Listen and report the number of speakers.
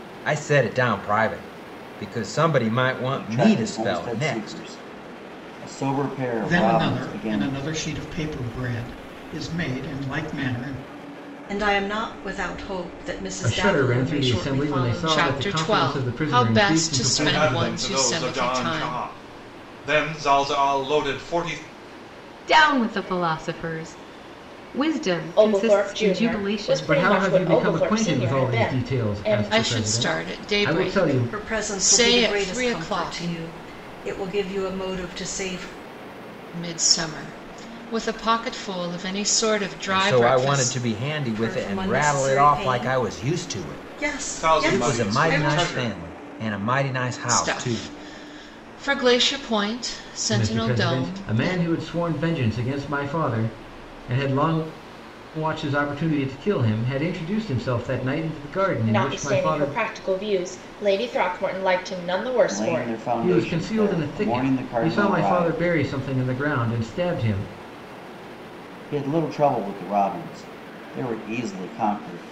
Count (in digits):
9